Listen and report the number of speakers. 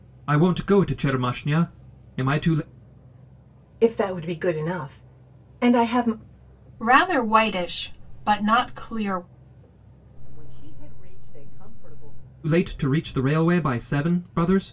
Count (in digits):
4